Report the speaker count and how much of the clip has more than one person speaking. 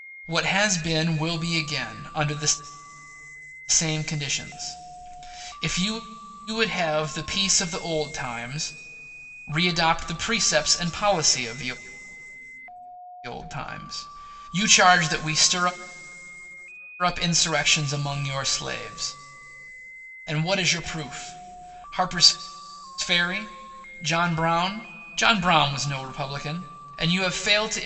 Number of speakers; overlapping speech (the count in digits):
1, no overlap